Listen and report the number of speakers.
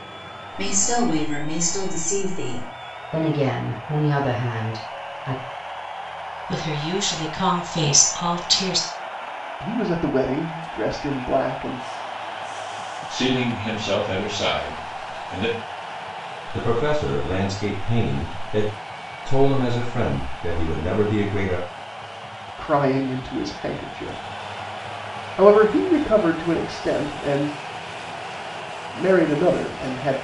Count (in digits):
6